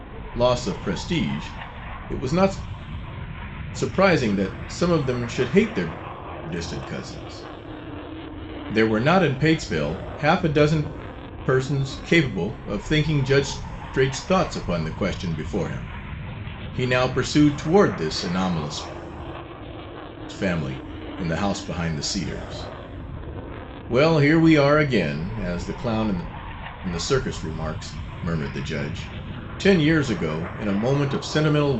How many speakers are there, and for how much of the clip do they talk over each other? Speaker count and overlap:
1, no overlap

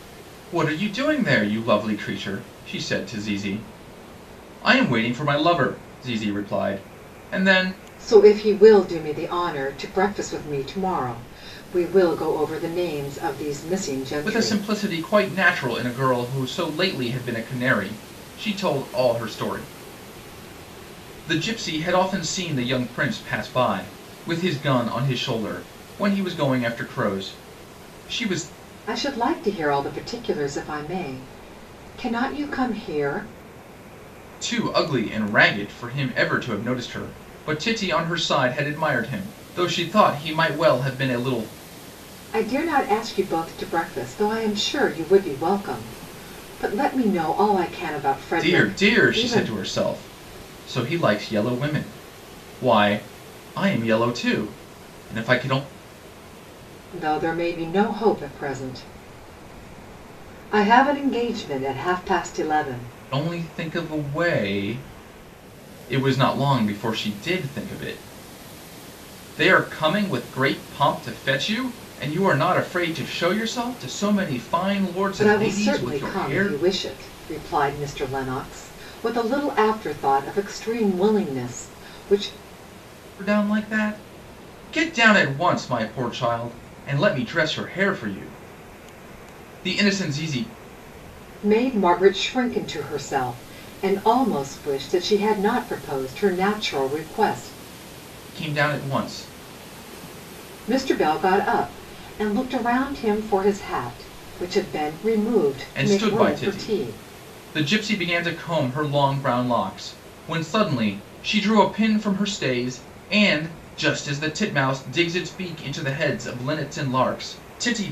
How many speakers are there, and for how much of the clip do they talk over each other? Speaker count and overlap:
2, about 4%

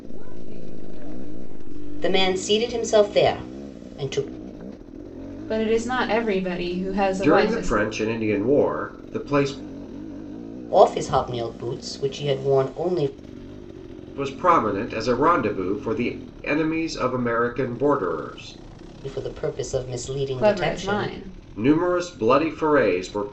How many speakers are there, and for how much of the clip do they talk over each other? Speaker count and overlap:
4, about 8%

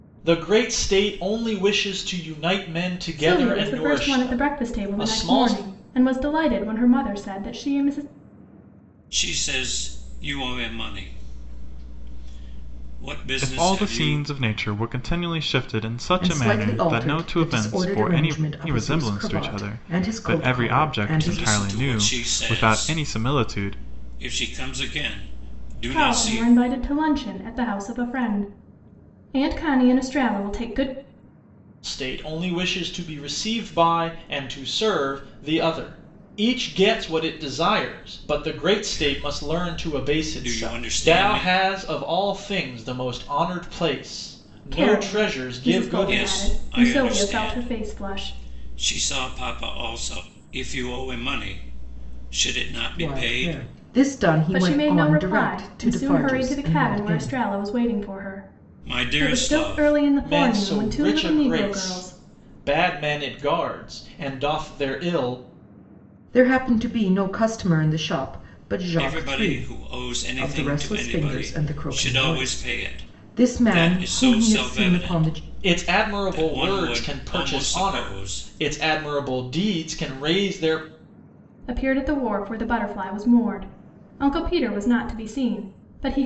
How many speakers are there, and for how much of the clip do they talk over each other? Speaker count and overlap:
5, about 37%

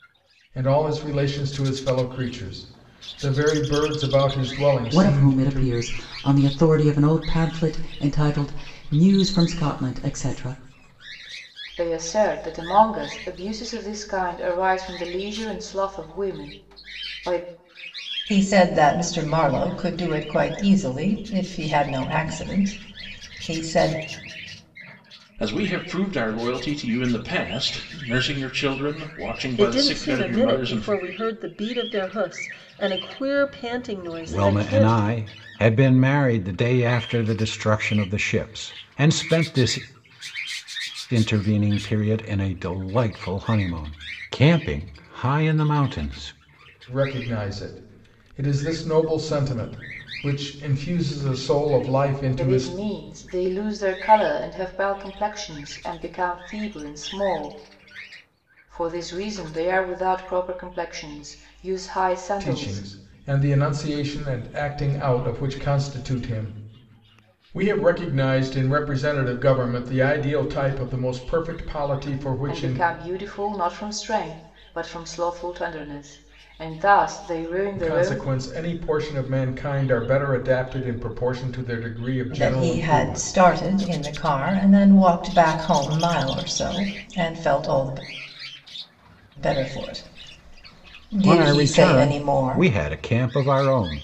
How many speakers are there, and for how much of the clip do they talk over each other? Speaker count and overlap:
7, about 8%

